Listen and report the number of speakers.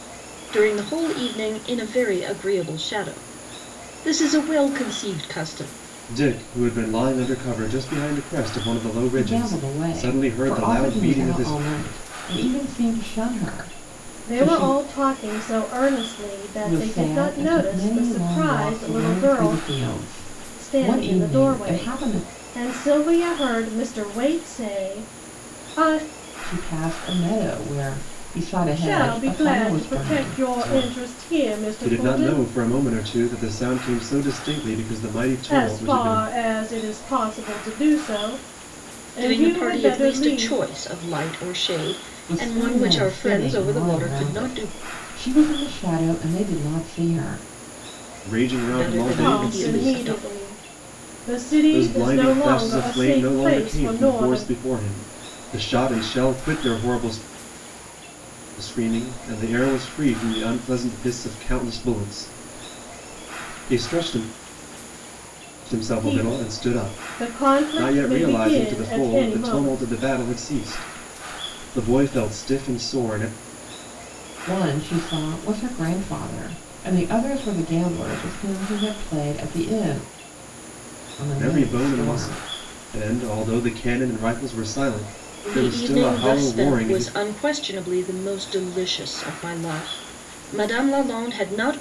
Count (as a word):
four